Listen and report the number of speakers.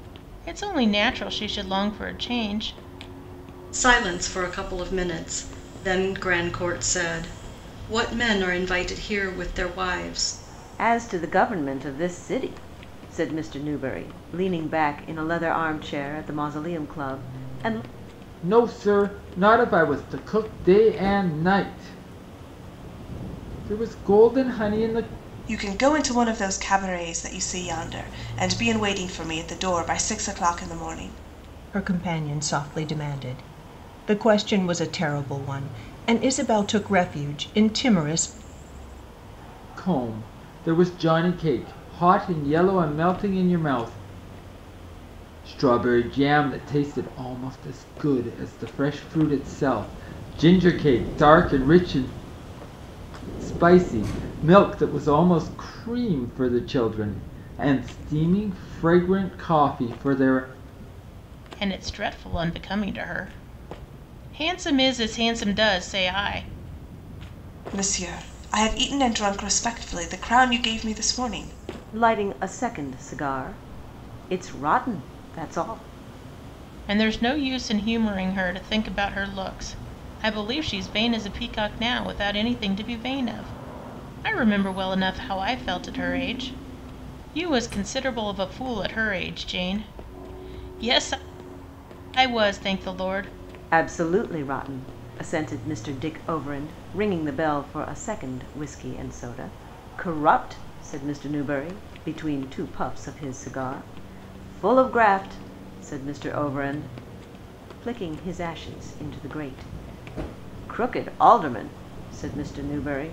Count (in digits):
6